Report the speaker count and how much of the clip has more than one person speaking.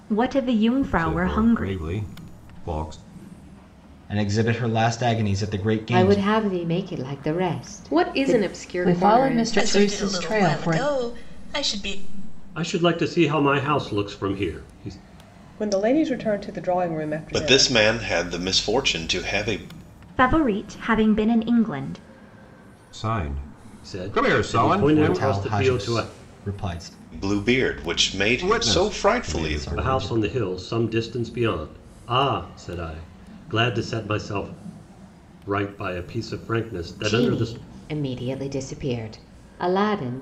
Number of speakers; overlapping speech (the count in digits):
10, about 22%